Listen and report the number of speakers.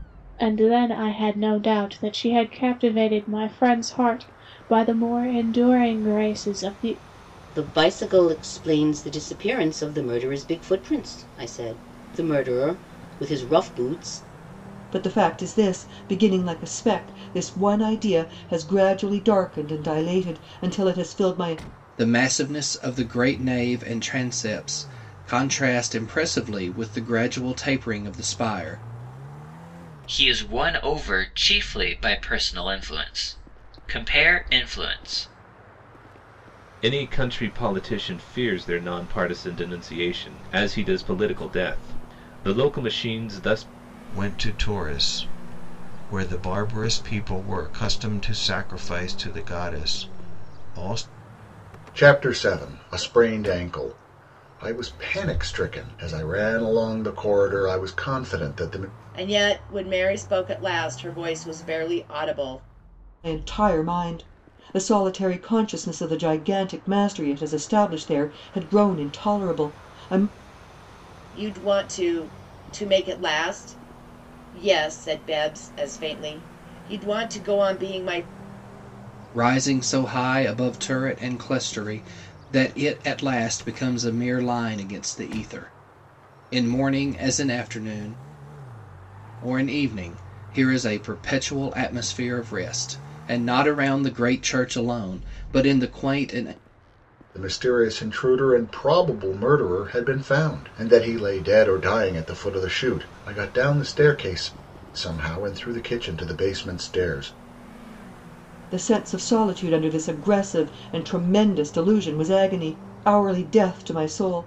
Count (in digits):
9